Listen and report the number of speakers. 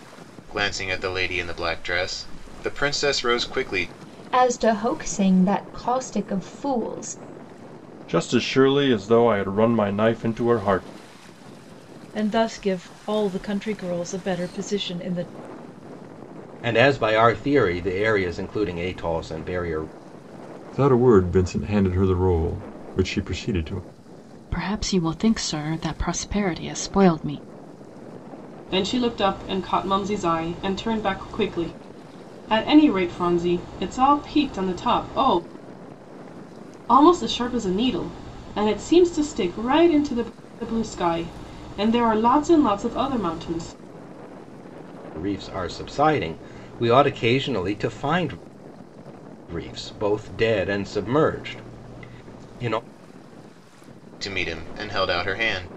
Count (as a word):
eight